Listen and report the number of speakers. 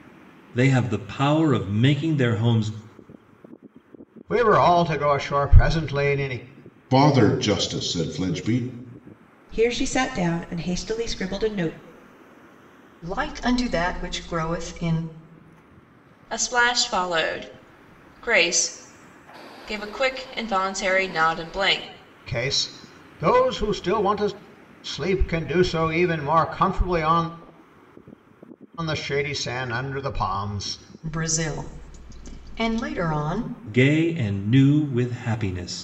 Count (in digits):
6